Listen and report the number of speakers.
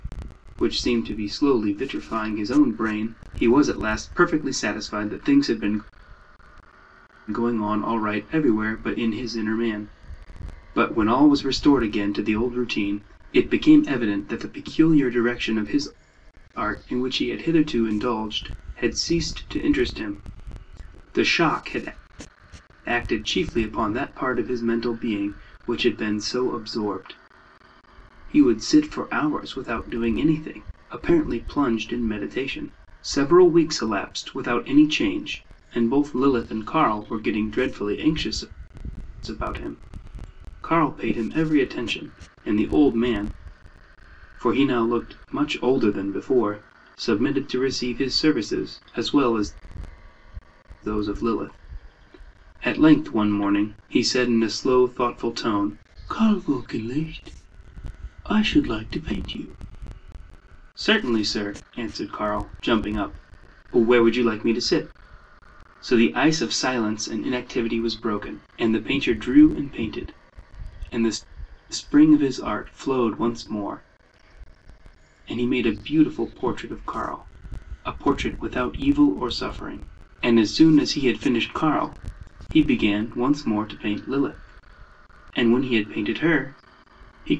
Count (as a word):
one